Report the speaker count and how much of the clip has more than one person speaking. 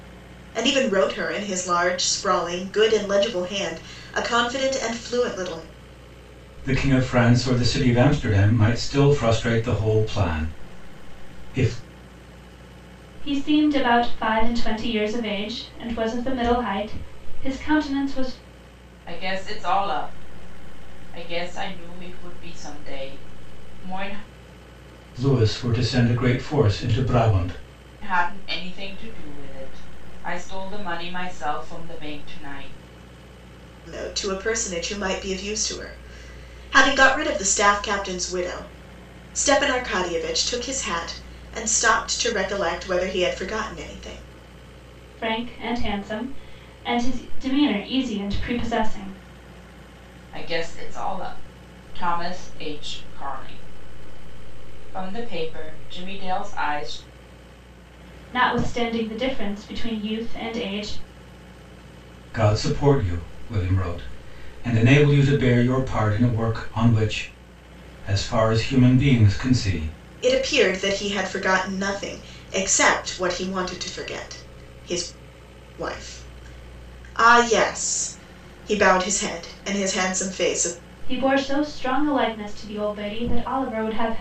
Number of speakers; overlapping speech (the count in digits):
4, no overlap